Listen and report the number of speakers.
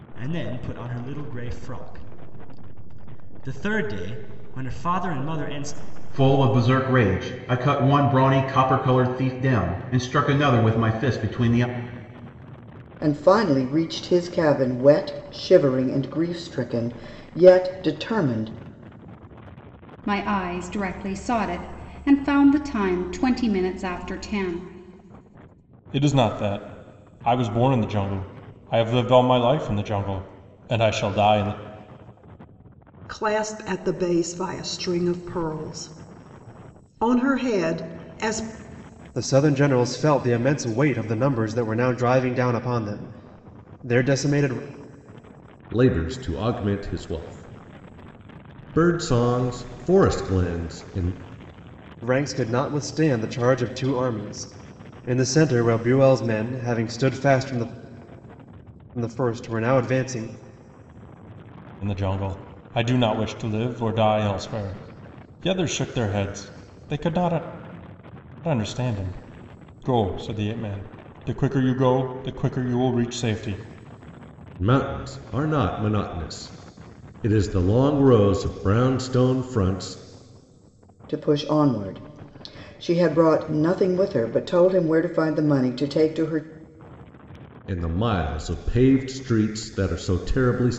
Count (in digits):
8